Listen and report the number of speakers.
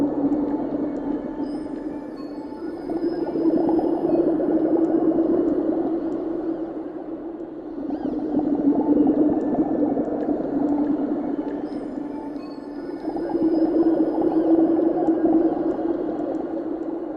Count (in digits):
0